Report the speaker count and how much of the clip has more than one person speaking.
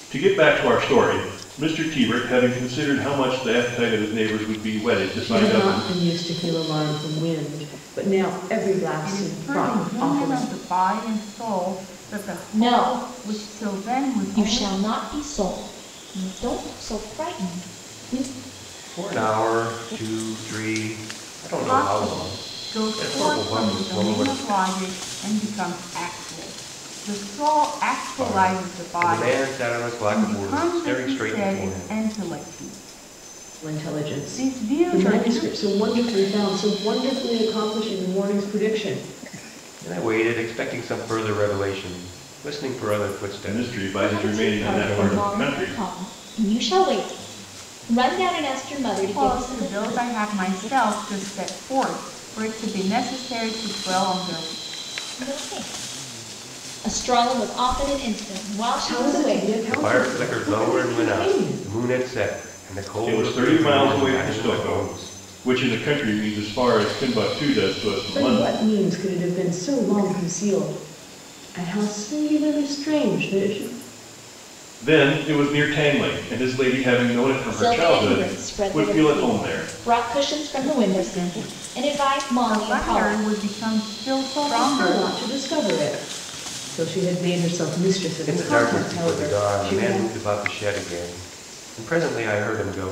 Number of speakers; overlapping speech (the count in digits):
5, about 30%